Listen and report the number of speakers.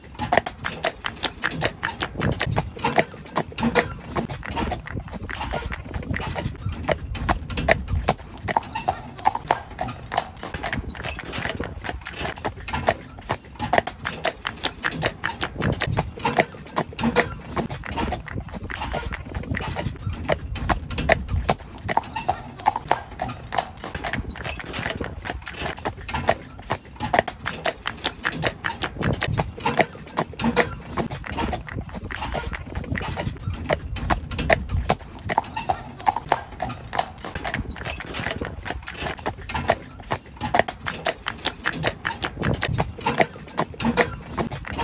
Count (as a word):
zero